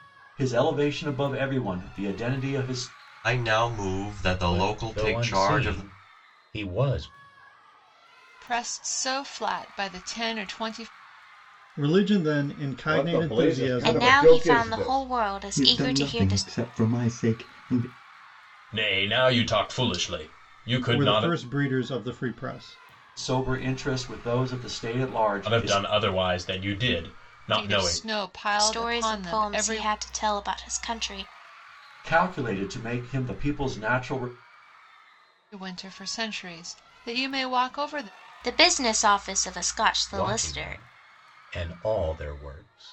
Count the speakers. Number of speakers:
9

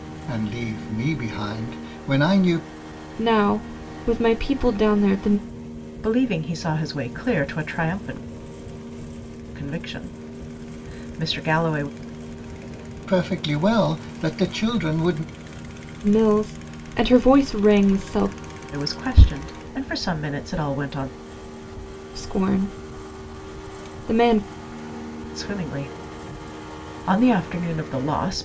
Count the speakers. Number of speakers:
3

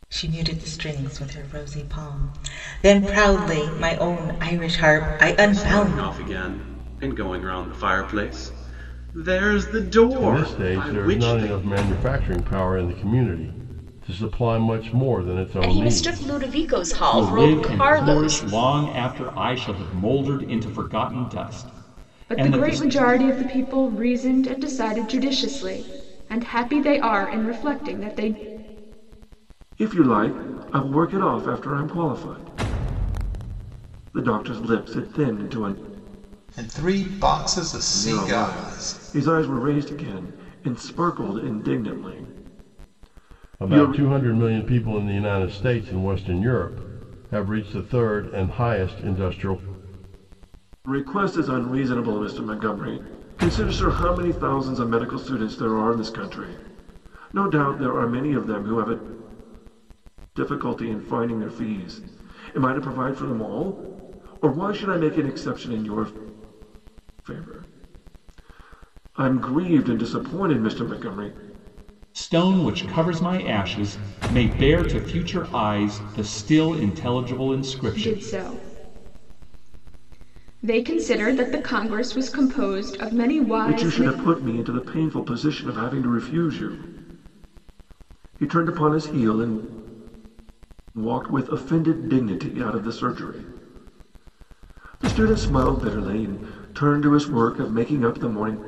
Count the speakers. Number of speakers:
8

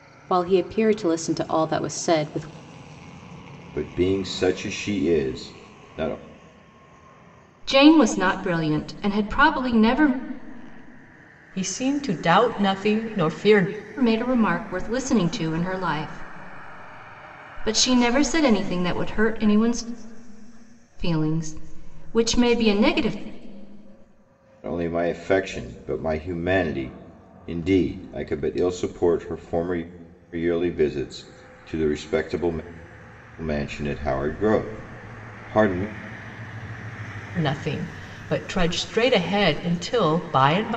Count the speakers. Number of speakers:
4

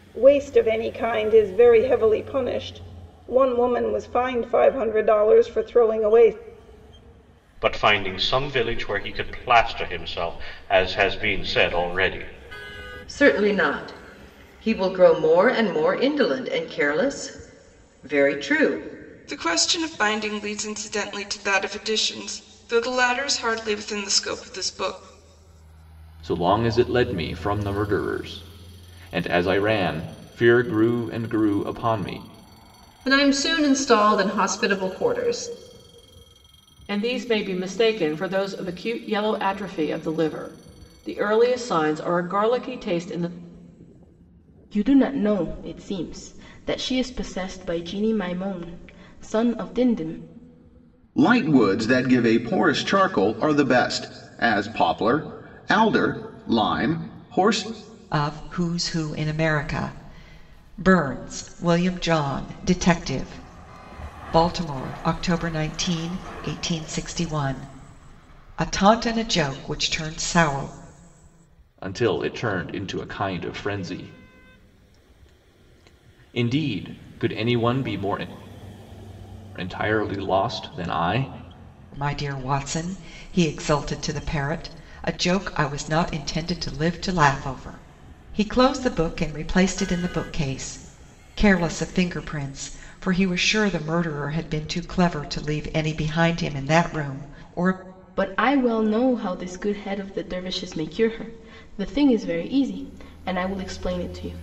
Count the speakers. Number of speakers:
10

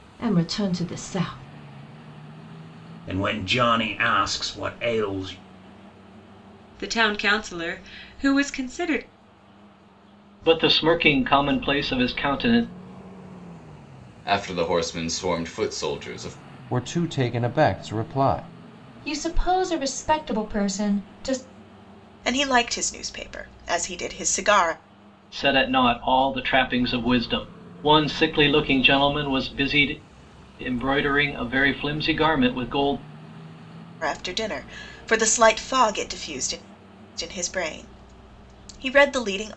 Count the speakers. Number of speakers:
8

